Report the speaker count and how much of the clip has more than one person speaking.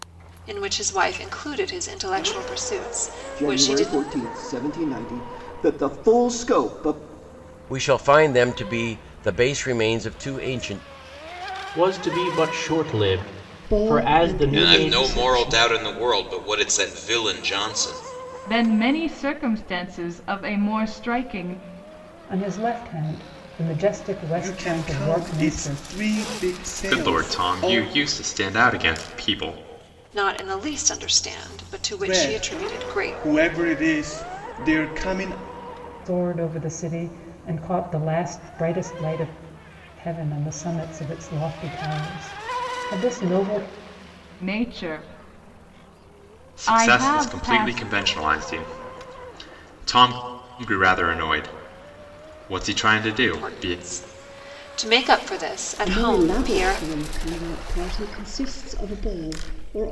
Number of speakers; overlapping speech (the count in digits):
10, about 16%